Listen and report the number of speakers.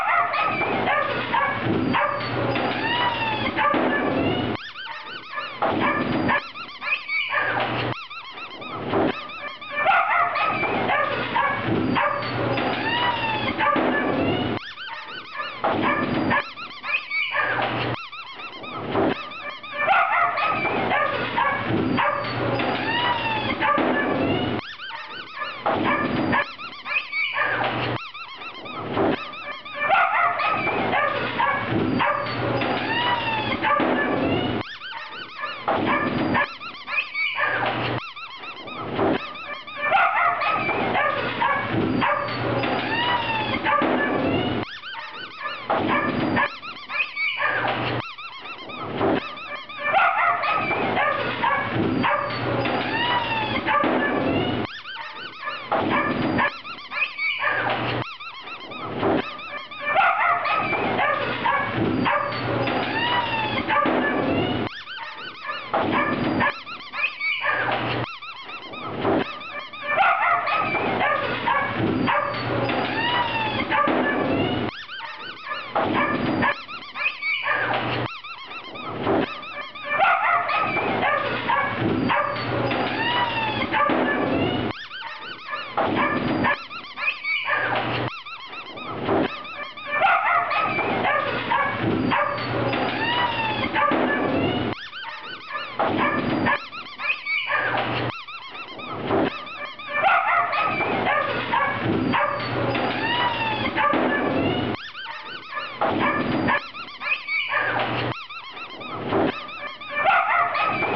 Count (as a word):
zero